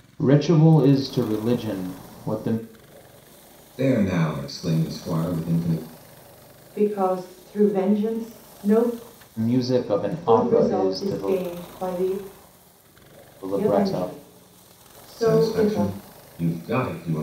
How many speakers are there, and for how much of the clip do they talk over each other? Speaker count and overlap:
three, about 14%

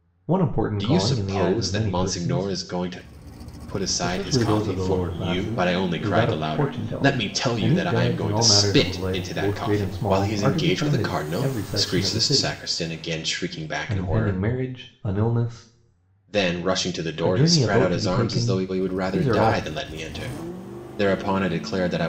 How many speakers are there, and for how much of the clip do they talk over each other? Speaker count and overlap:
two, about 60%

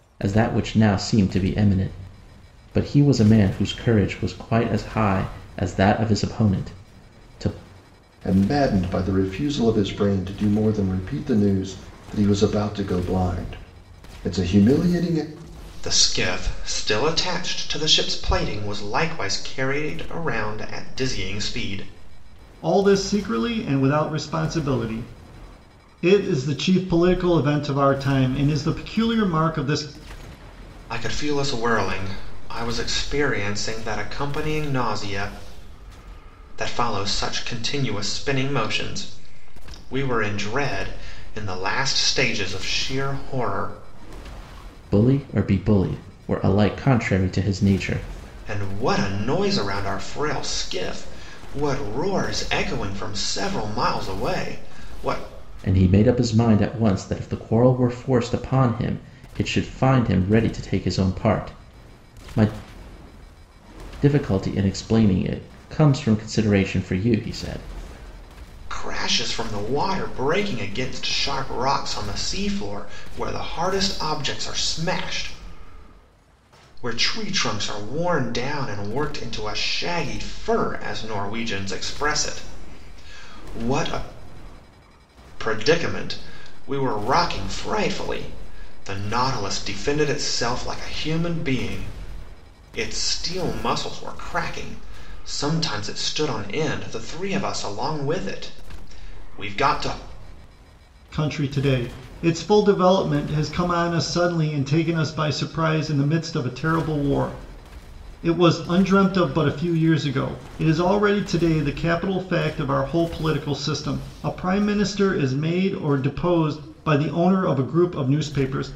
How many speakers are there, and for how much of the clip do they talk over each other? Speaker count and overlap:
four, no overlap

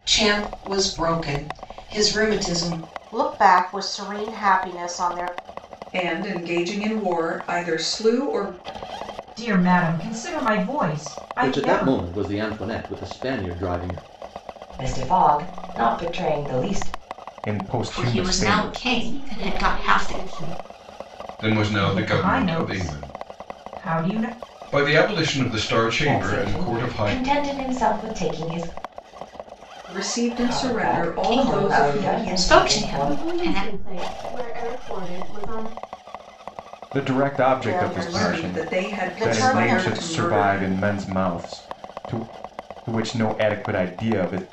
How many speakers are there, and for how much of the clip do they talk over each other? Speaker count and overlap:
ten, about 27%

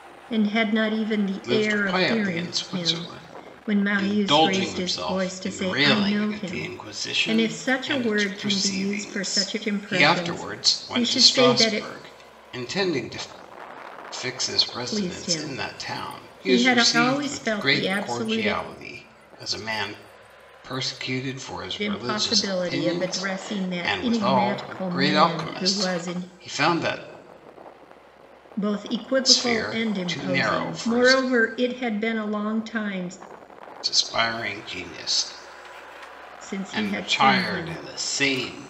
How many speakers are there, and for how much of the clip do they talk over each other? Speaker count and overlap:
two, about 53%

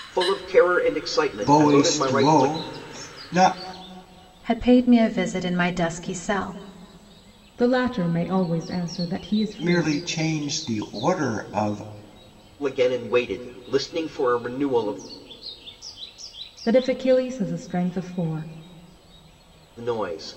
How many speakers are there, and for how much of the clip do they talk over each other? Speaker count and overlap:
four, about 7%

